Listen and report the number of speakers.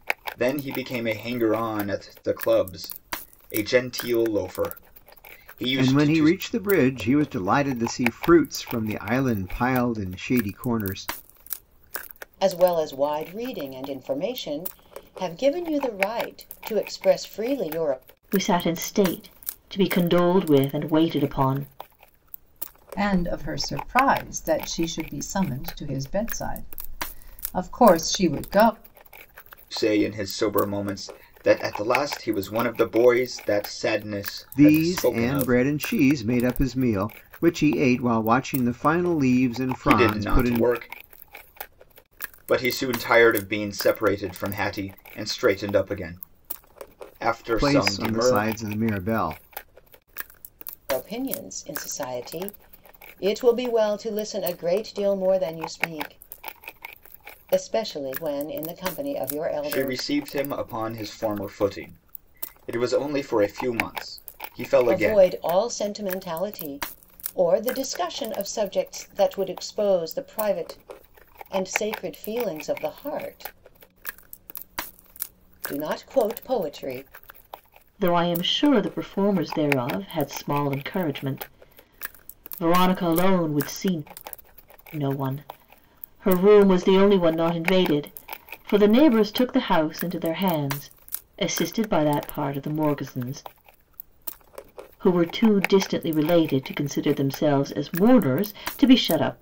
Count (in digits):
5